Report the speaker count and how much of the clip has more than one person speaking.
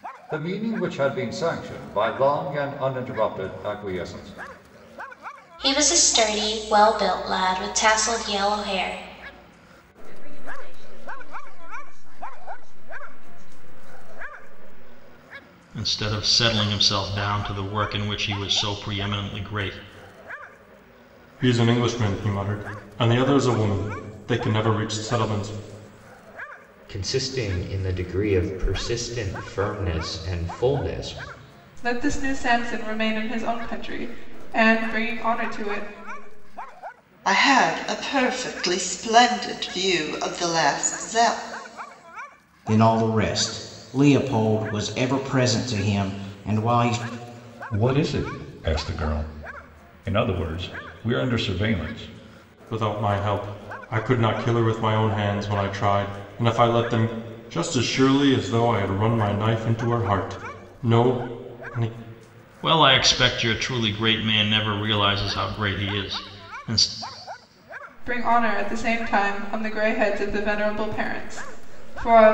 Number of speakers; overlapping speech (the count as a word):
ten, no overlap